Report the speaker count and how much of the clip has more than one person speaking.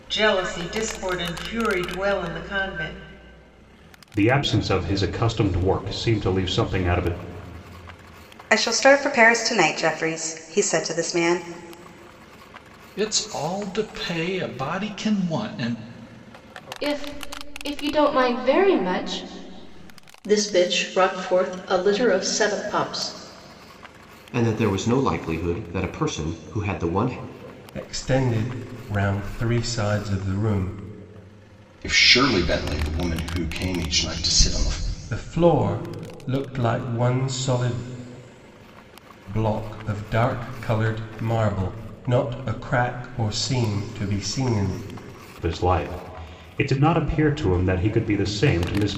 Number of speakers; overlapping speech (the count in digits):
9, no overlap